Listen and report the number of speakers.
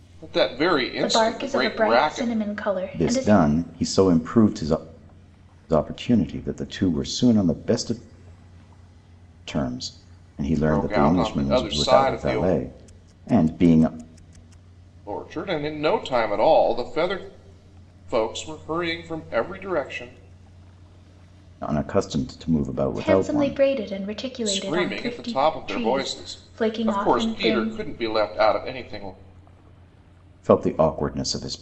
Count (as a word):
three